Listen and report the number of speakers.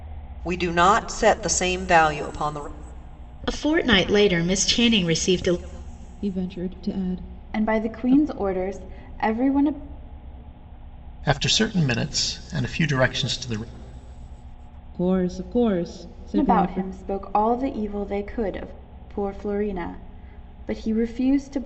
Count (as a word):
five